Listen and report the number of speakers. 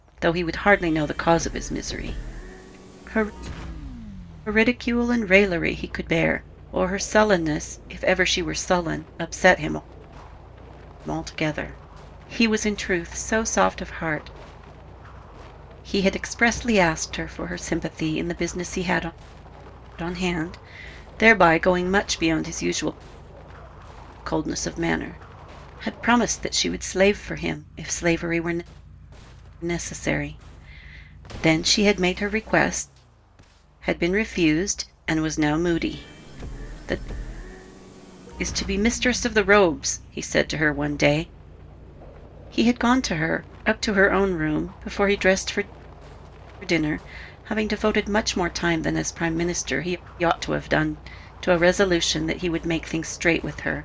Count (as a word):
one